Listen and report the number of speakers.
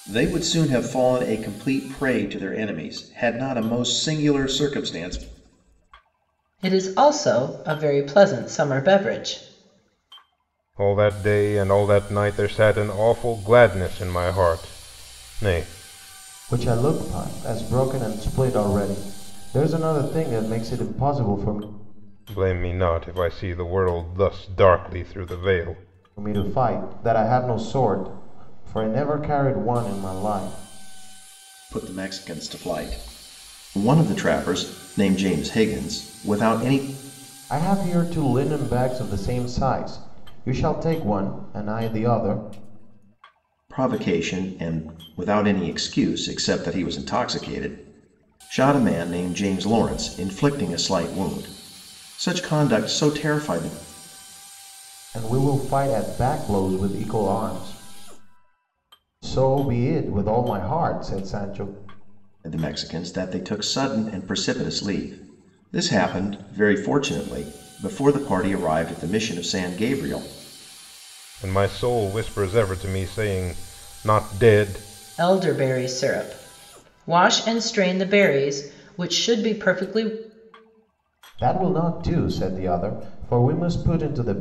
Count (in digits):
4